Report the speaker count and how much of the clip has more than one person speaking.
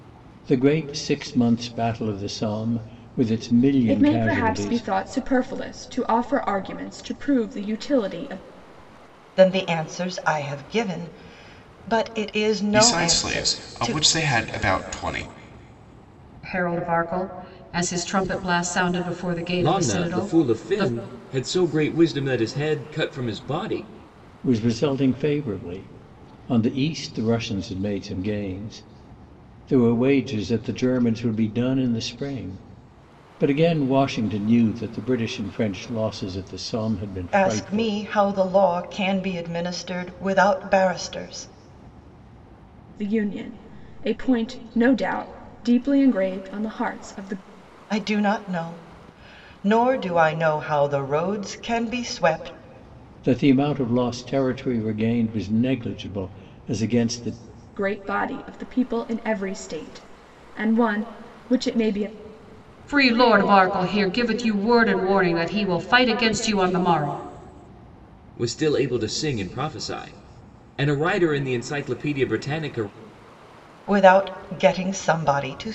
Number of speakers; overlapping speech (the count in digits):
6, about 6%